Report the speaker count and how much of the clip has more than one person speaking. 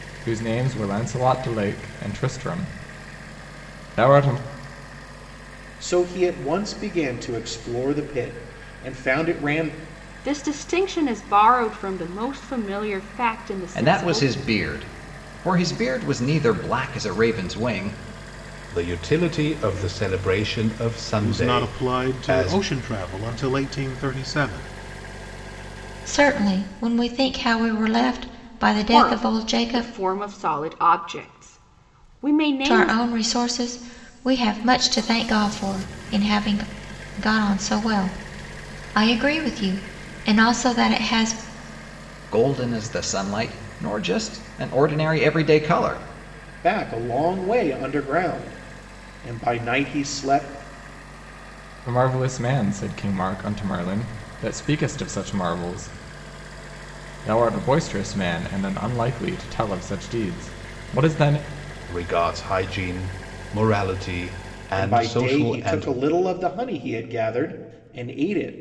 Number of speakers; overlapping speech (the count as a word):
seven, about 7%